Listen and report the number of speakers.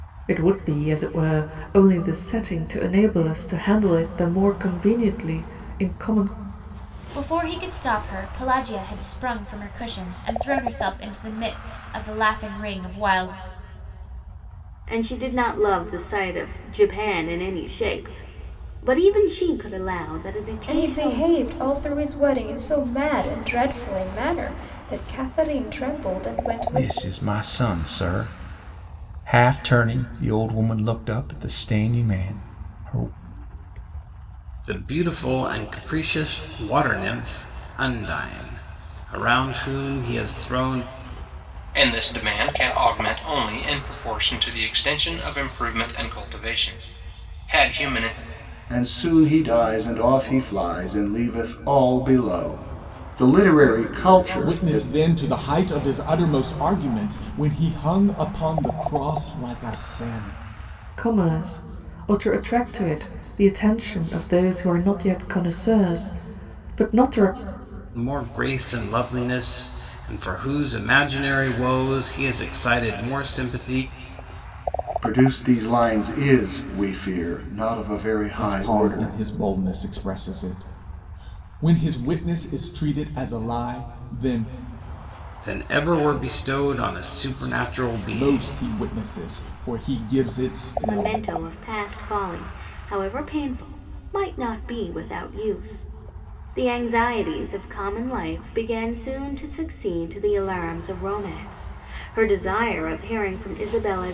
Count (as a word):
nine